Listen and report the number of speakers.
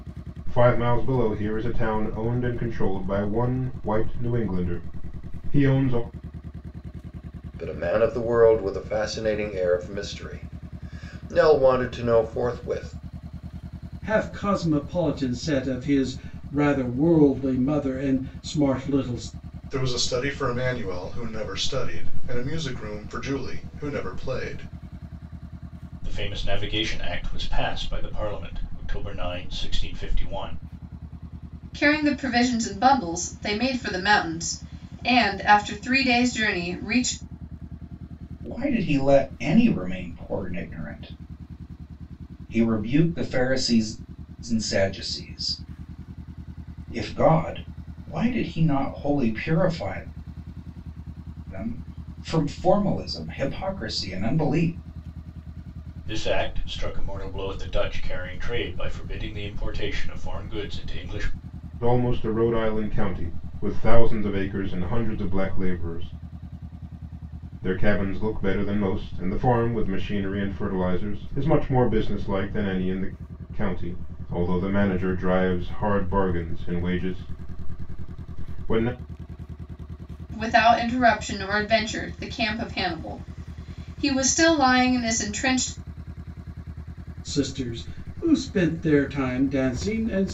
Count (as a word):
seven